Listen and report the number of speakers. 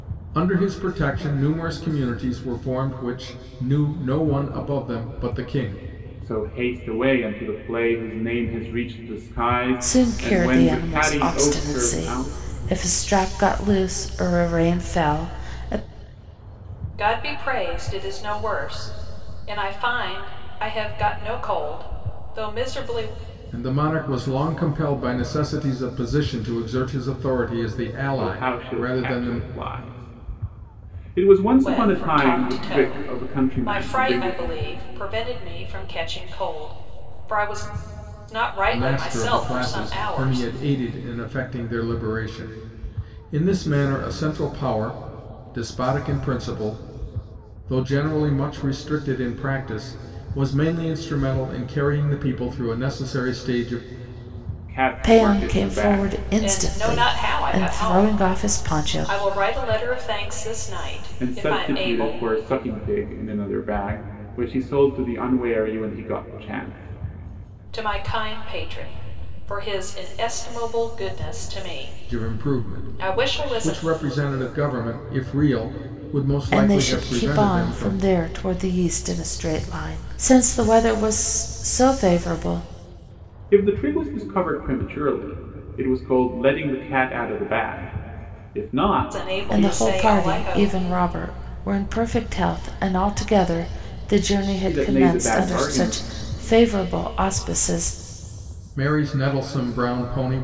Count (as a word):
four